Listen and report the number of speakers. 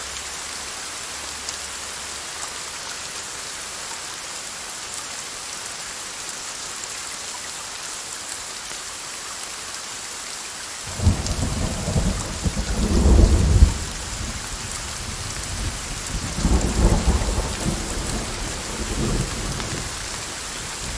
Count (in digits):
0